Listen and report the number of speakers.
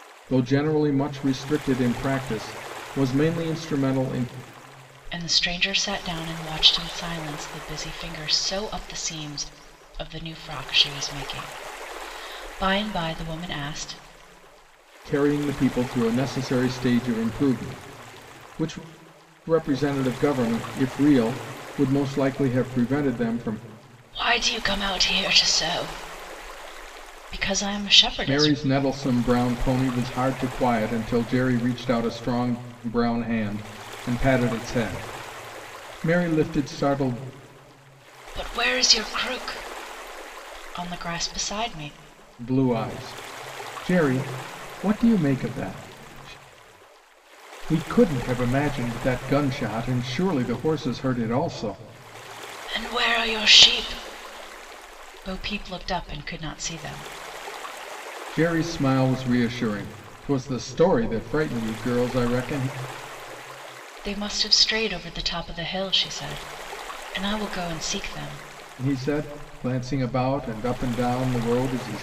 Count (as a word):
two